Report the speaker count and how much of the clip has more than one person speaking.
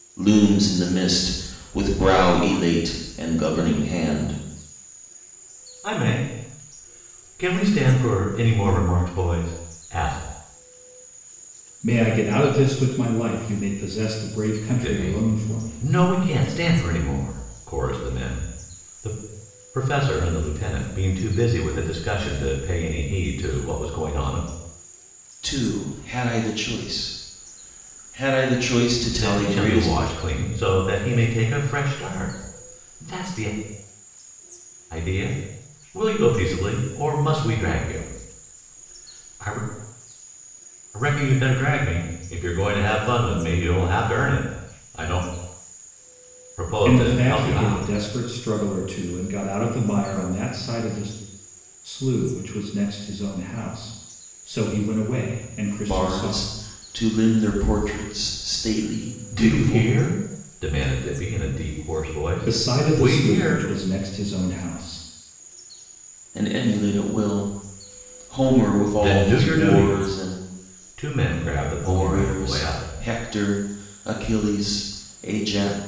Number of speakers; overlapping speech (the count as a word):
three, about 11%